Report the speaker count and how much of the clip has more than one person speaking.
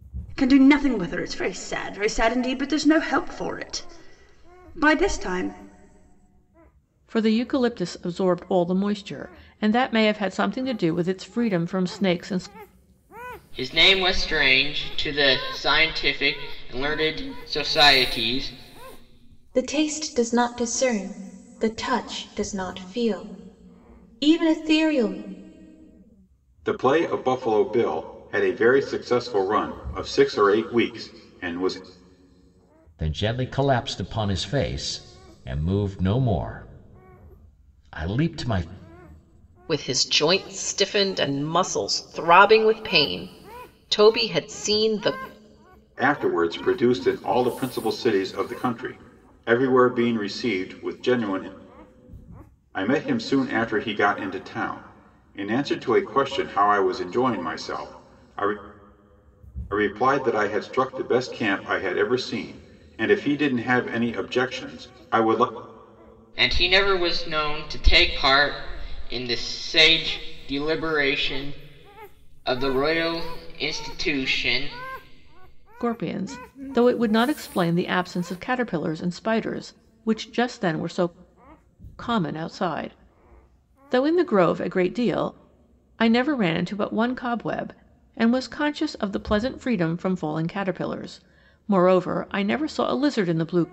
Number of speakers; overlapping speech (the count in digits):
7, no overlap